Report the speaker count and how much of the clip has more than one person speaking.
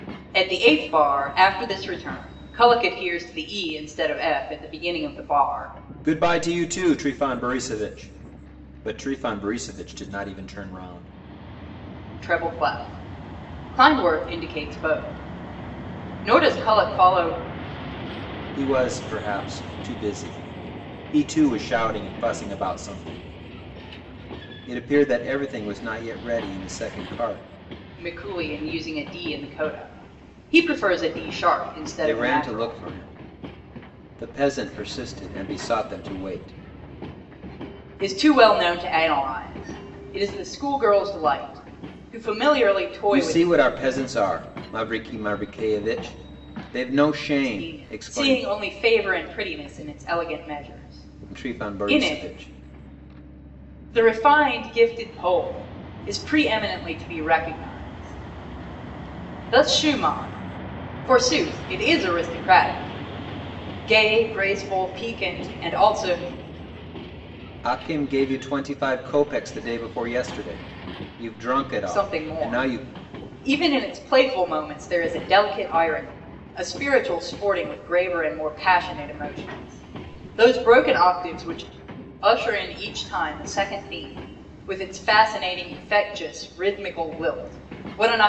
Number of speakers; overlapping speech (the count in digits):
2, about 5%